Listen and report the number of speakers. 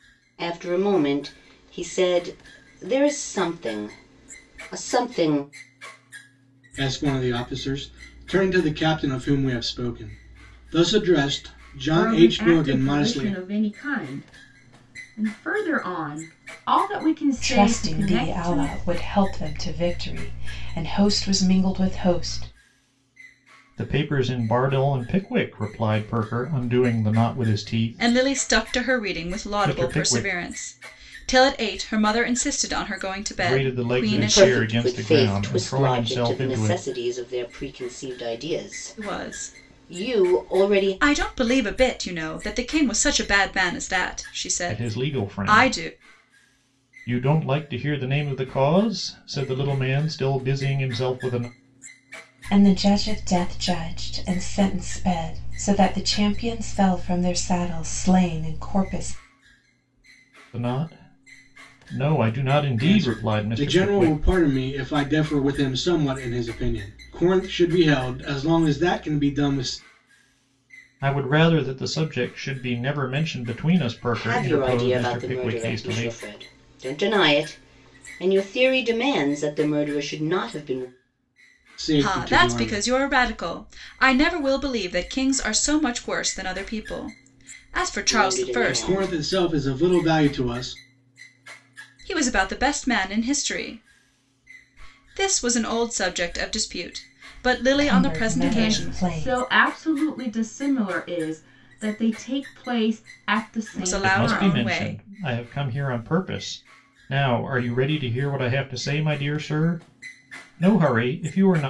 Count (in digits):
6